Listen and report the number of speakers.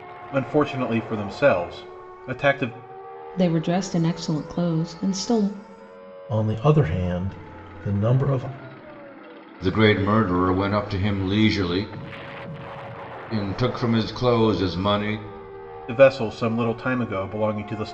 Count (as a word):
four